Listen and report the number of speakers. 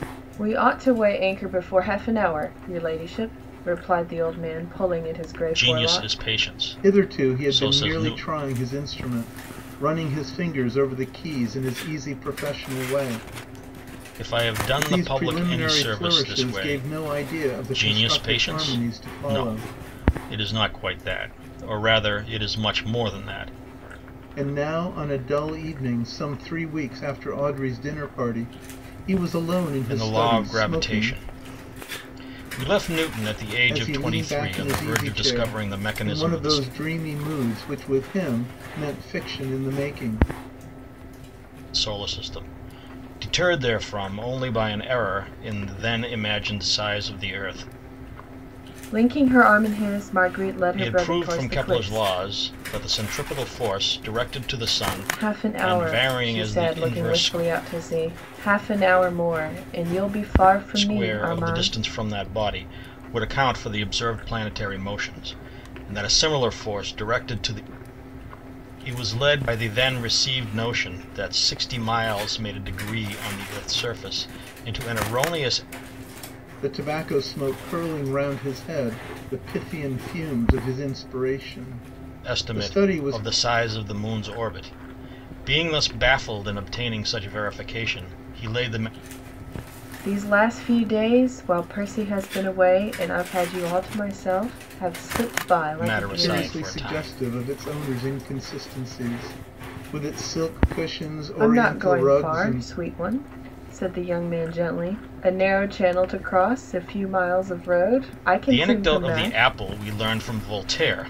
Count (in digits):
3